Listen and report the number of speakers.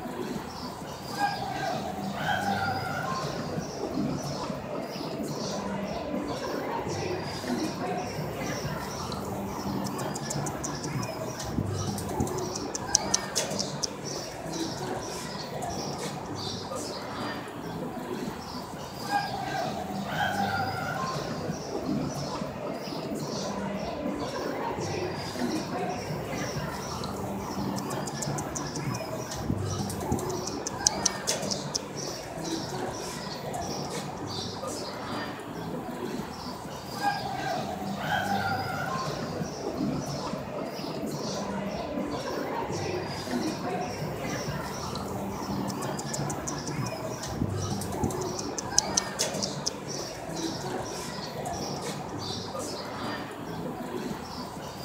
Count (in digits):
0